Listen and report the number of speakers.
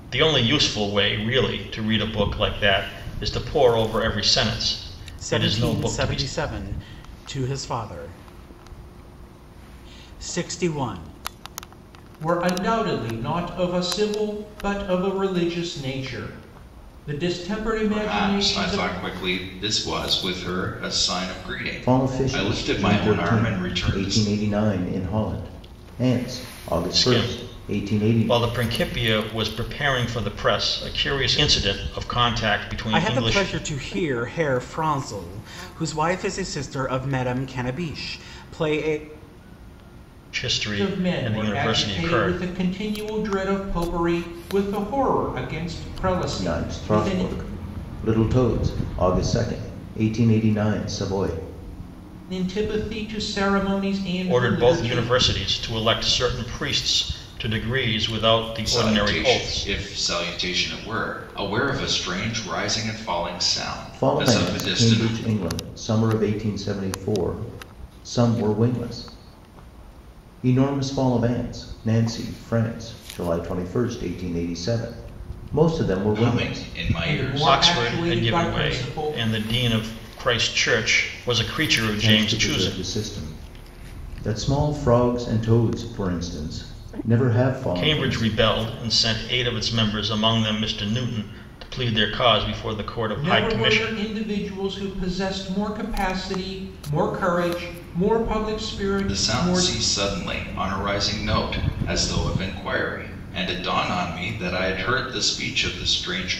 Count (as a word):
five